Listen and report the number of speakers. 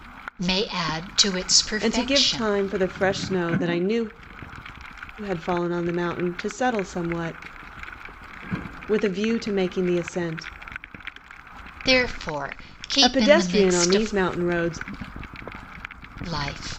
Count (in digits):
2